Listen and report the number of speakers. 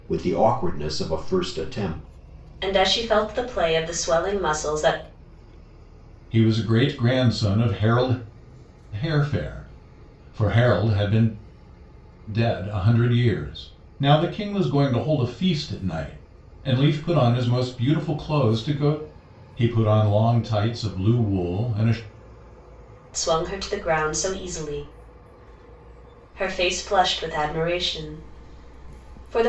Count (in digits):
3